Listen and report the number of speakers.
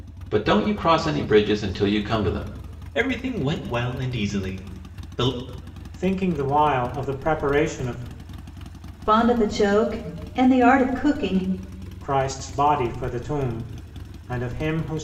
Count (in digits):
4